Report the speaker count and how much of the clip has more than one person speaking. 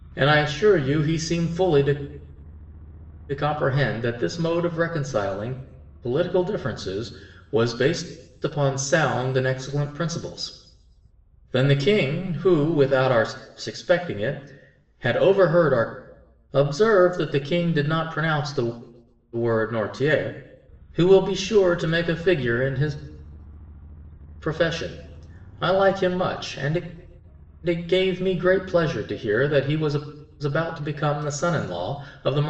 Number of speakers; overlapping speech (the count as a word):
one, no overlap